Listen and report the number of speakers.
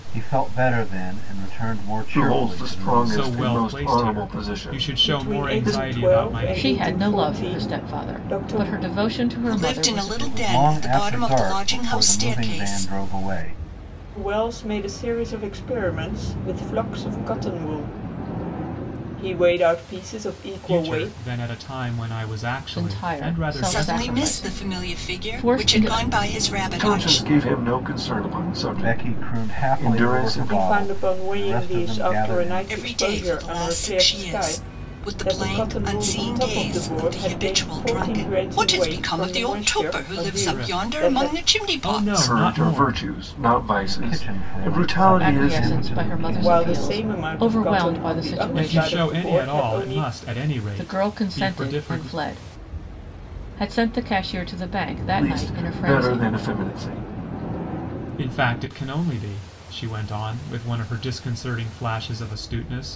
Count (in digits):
6